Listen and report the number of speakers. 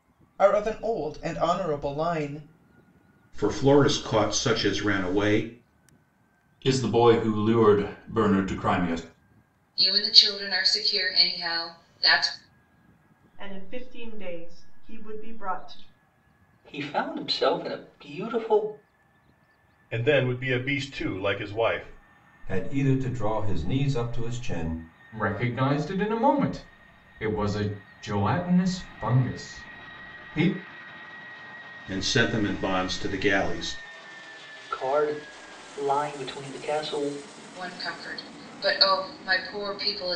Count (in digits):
9